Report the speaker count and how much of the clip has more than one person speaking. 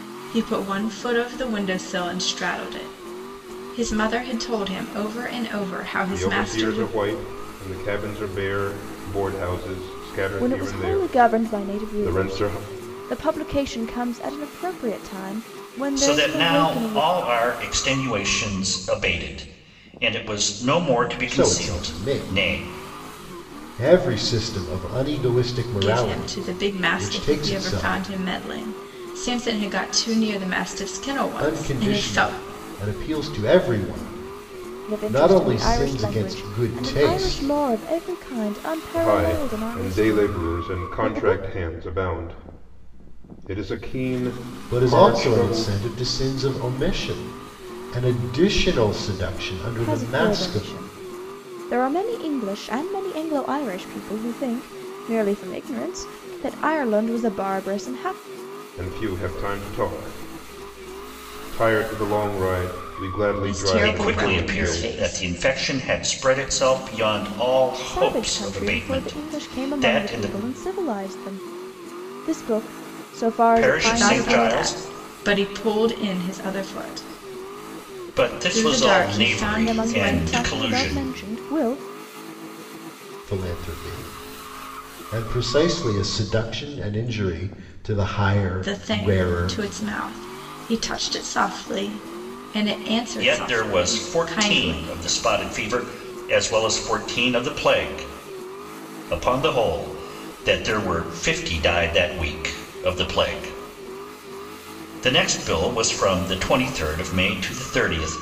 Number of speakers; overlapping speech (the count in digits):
5, about 26%